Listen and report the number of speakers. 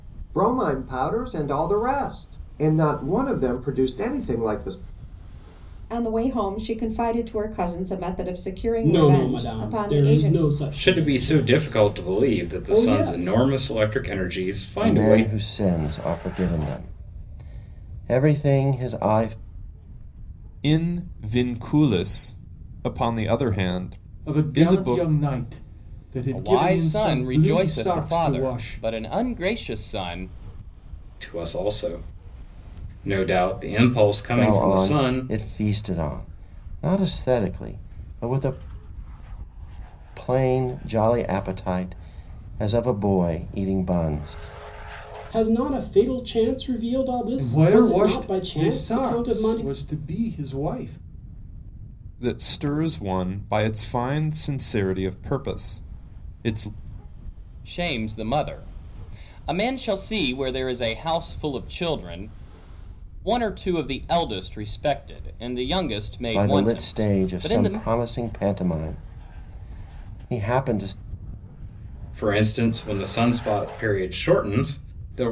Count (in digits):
8